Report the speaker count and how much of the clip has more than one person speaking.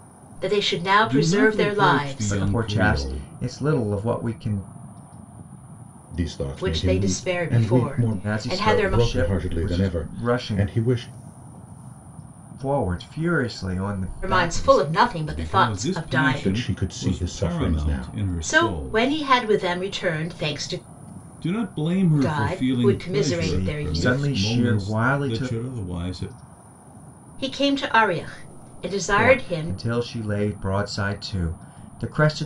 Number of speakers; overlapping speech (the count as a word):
four, about 45%